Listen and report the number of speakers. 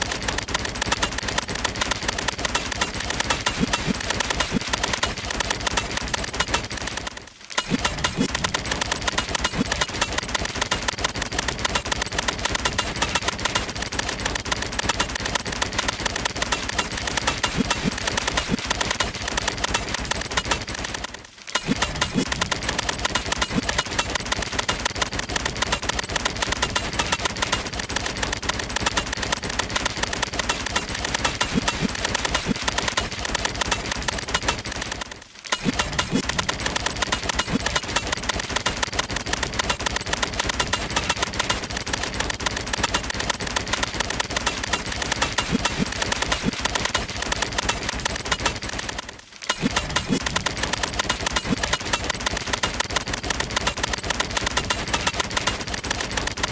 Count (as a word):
zero